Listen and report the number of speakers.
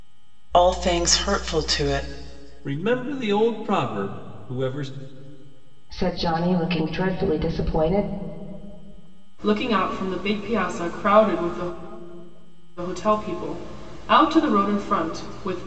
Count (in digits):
4